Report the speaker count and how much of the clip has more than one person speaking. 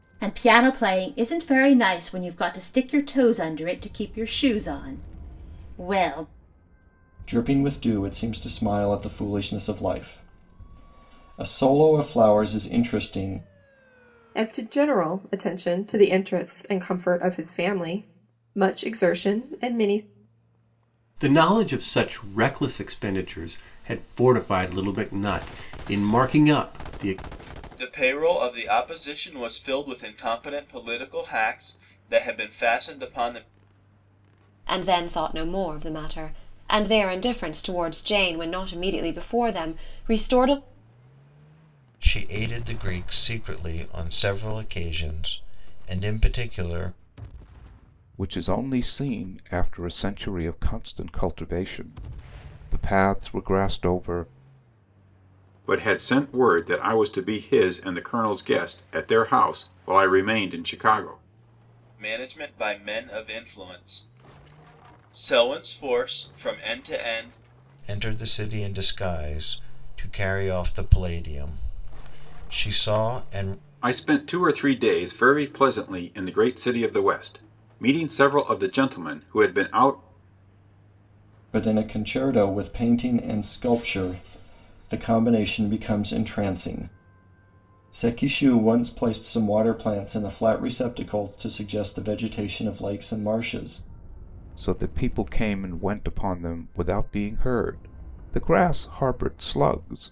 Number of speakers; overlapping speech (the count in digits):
9, no overlap